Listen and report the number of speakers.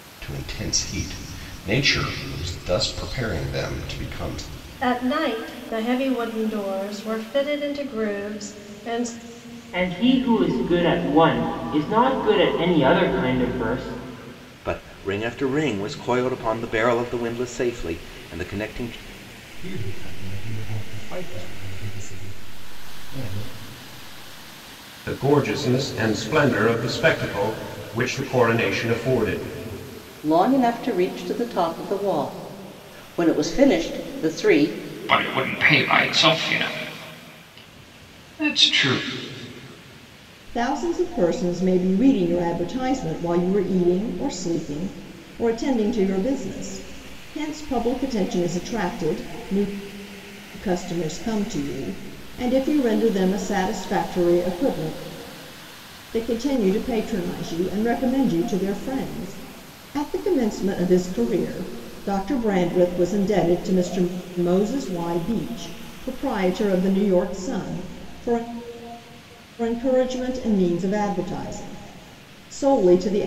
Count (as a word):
nine